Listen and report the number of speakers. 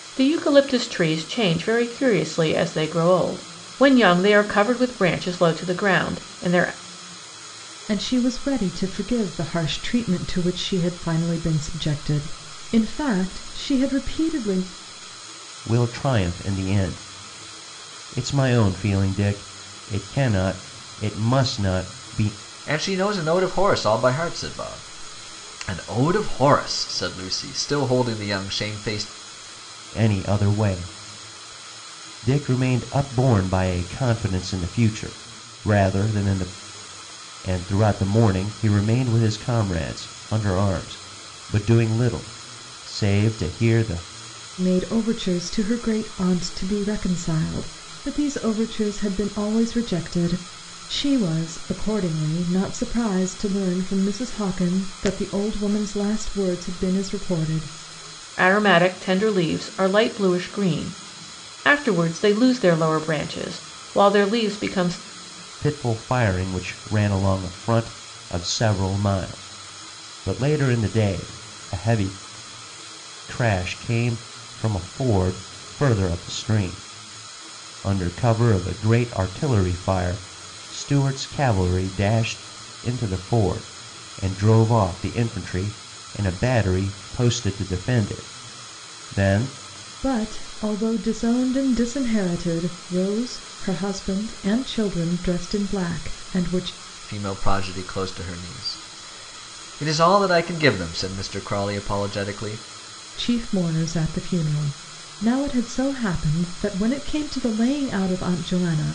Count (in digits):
4